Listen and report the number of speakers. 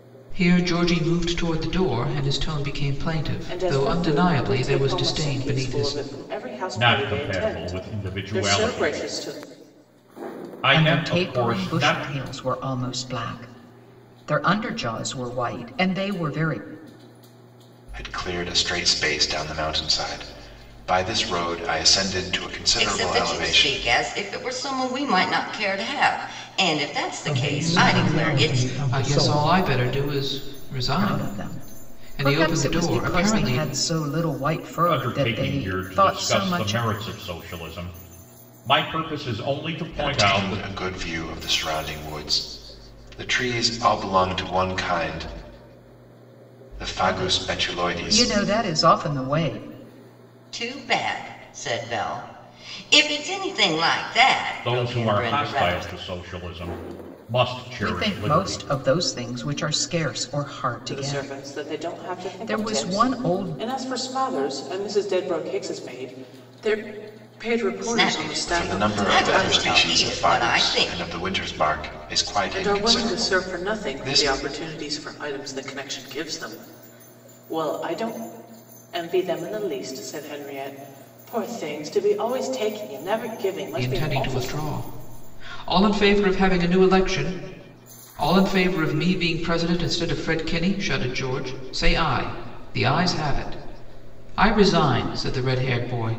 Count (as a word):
seven